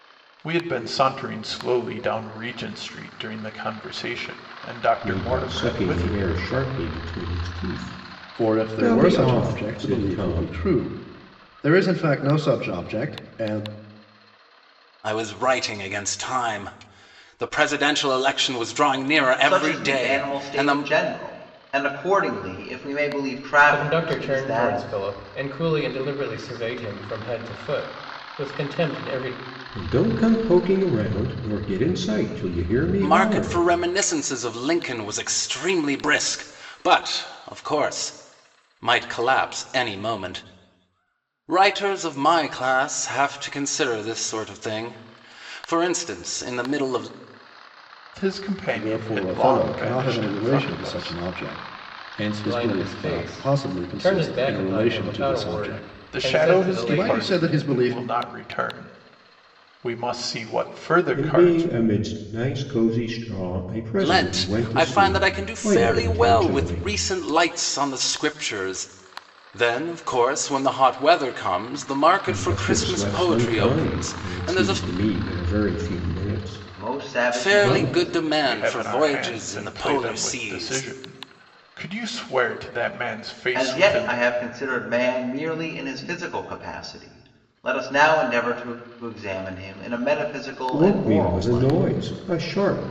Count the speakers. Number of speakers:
six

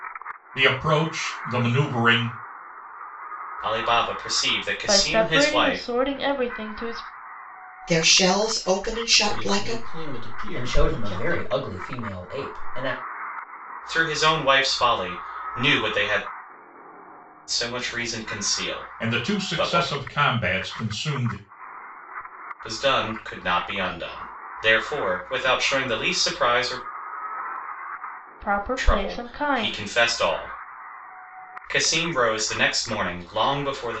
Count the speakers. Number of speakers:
six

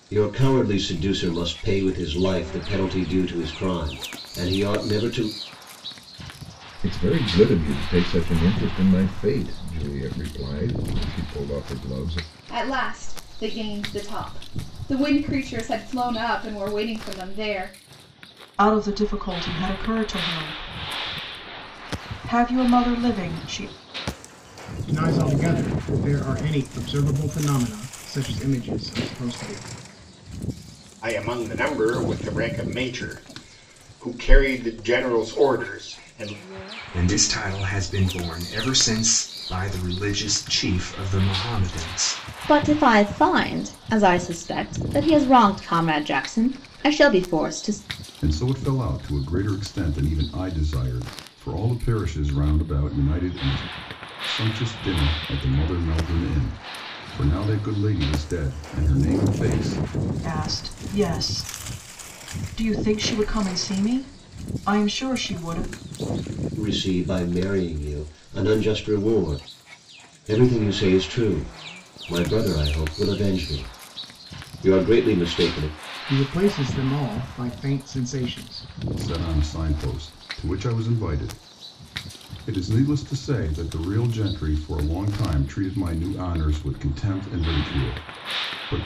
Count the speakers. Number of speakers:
nine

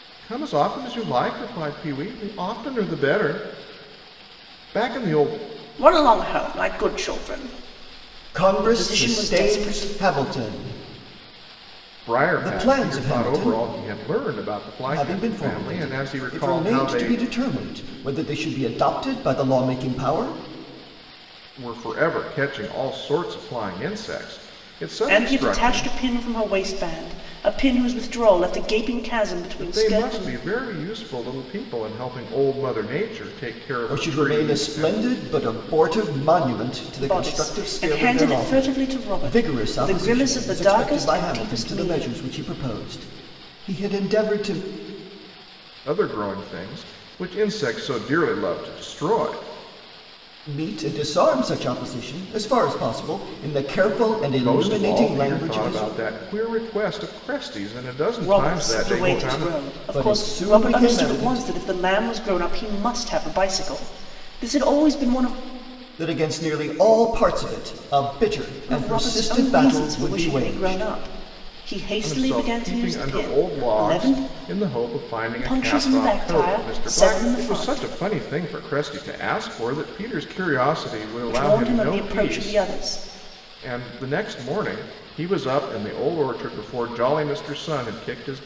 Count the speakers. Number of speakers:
three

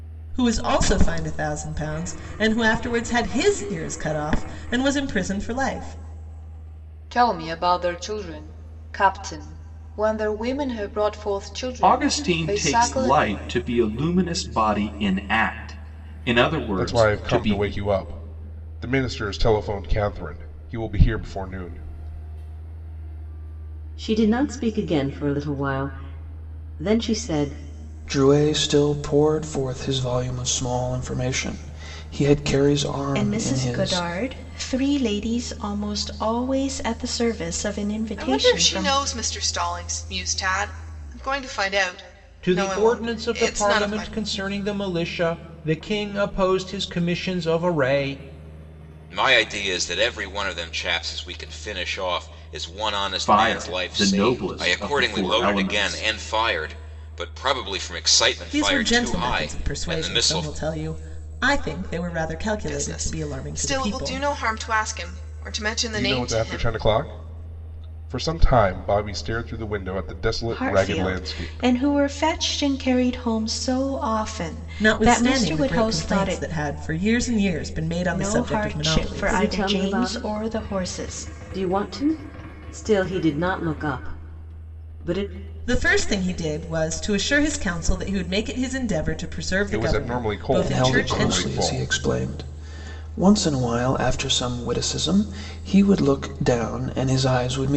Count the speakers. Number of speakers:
ten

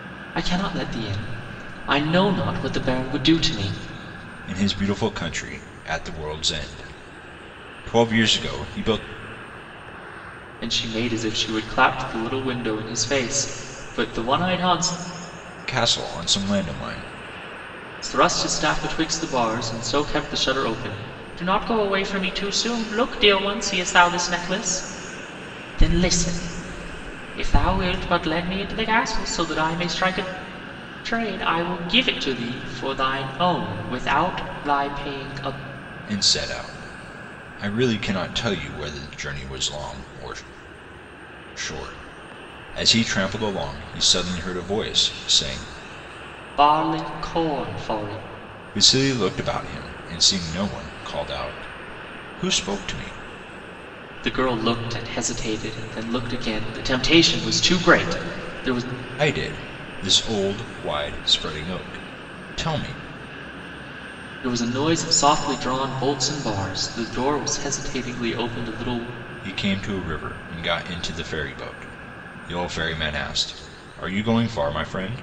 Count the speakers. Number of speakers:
two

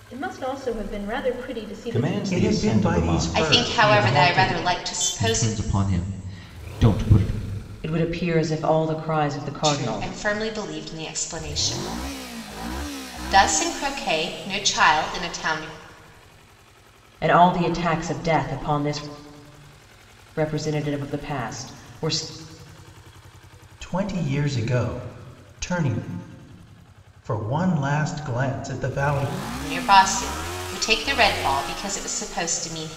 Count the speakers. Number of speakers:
six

